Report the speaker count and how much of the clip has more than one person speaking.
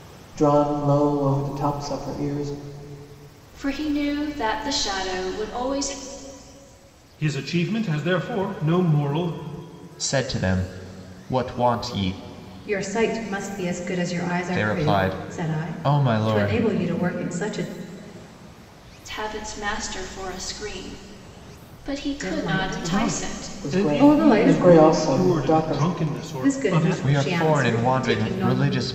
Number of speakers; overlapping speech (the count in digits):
5, about 27%